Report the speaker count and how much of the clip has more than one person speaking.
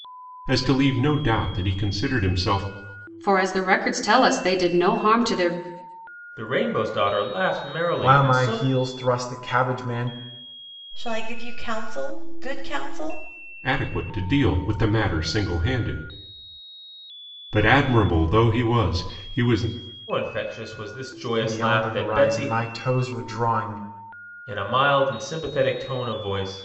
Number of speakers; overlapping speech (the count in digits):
5, about 7%